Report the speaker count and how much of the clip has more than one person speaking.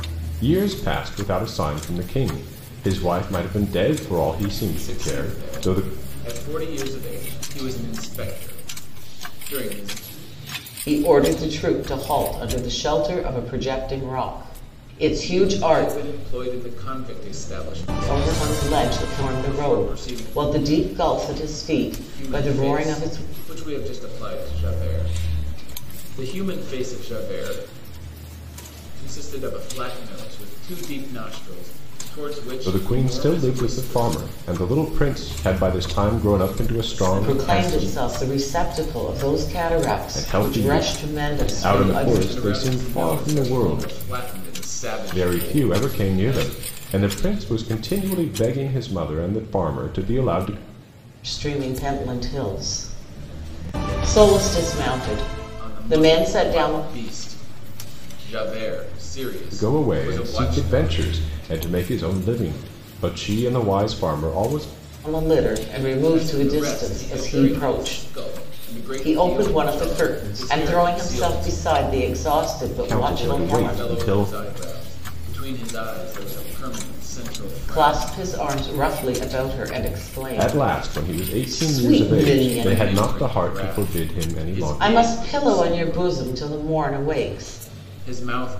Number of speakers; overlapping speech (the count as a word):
three, about 33%